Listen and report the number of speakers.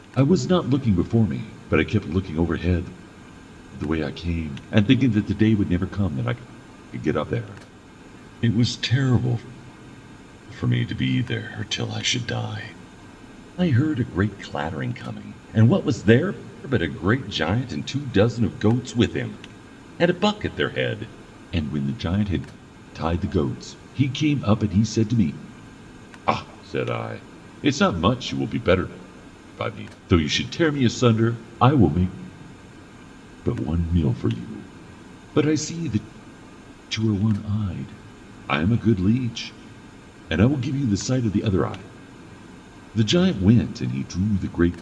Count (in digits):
1